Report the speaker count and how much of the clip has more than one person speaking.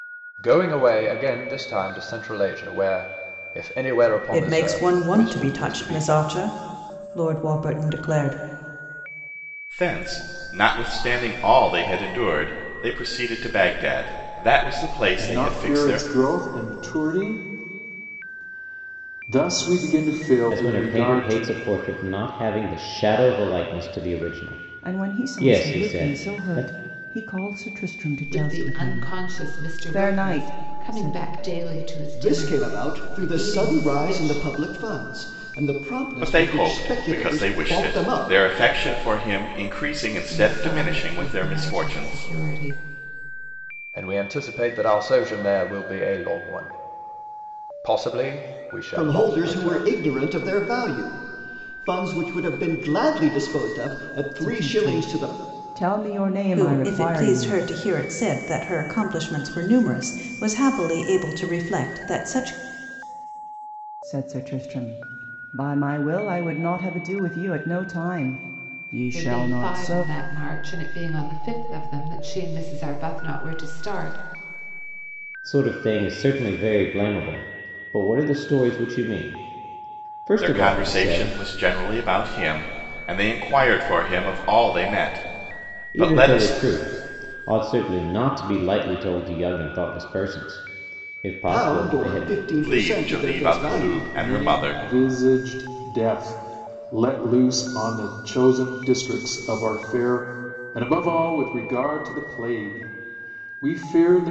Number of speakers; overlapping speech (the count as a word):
eight, about 24%